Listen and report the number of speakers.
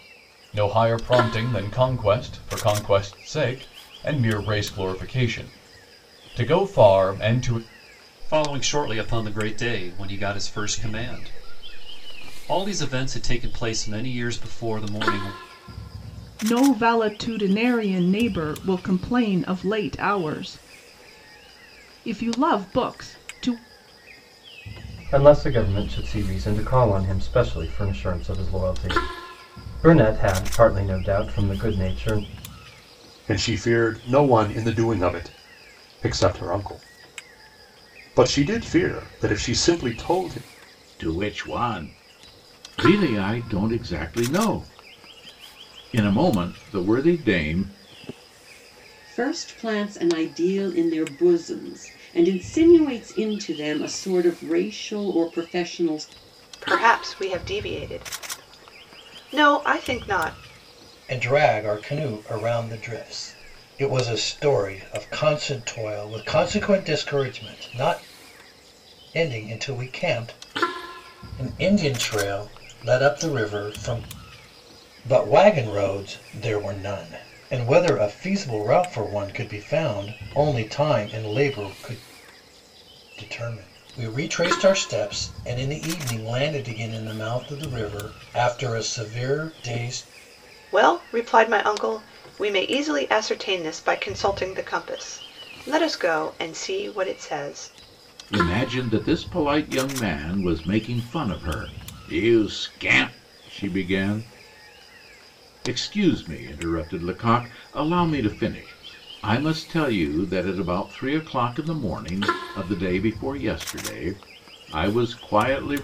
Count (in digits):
9